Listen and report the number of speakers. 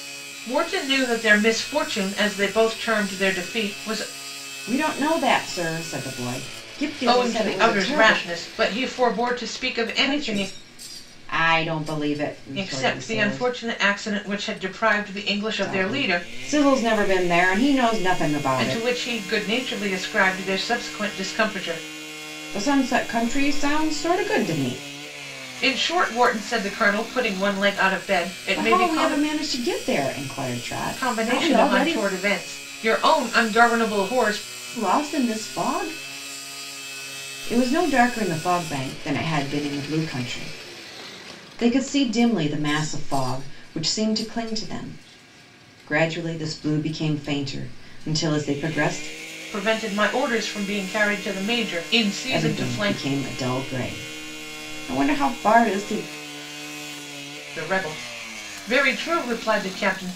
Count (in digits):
2